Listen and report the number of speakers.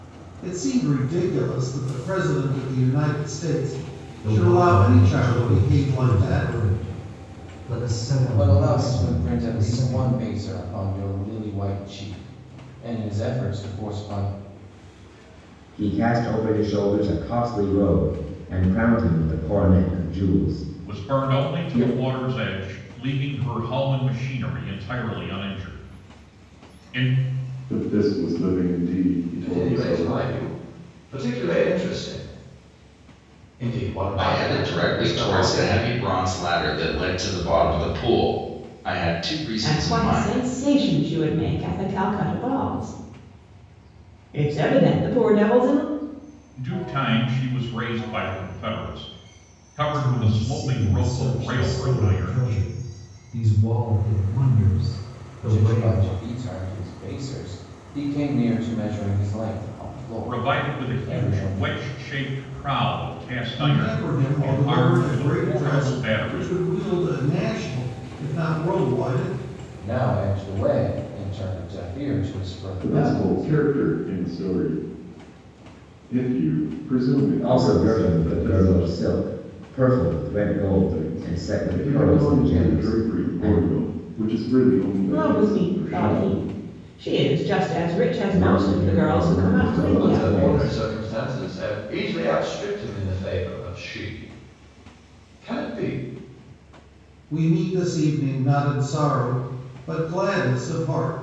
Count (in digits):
9